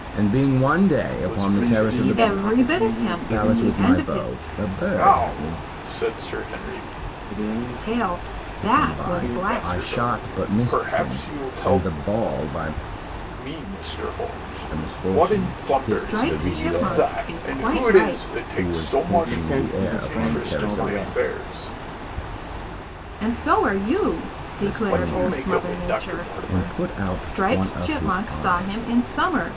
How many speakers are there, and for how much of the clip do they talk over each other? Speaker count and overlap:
4, about 64%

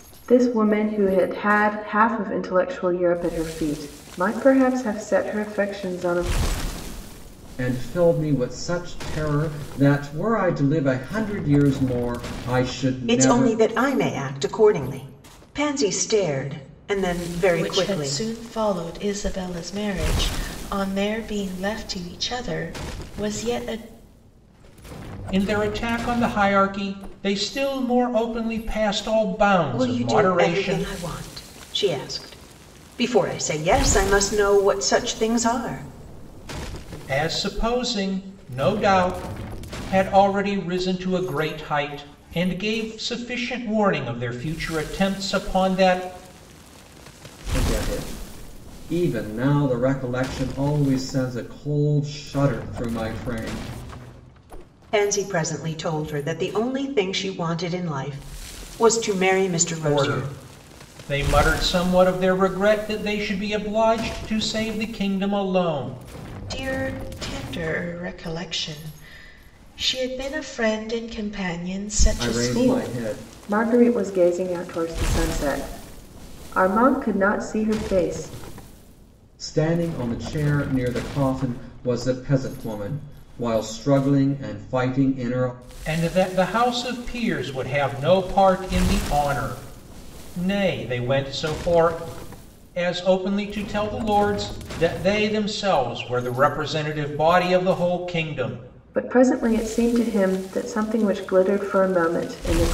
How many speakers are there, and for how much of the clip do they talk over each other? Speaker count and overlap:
5, about 4%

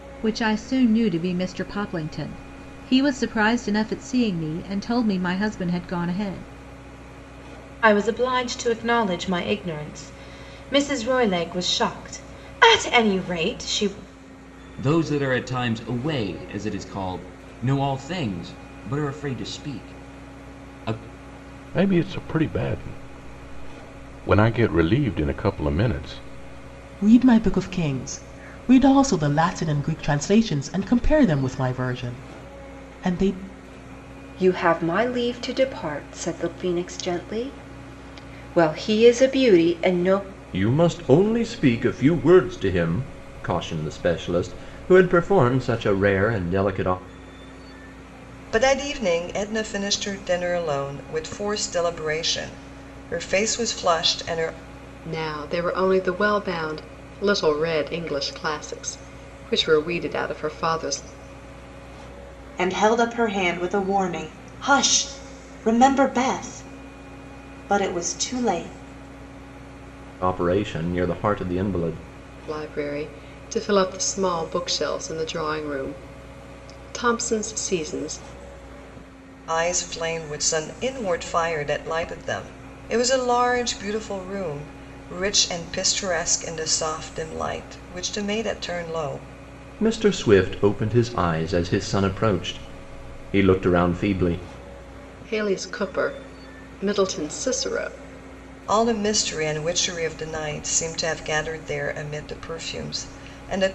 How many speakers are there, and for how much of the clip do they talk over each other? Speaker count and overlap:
10, no overlap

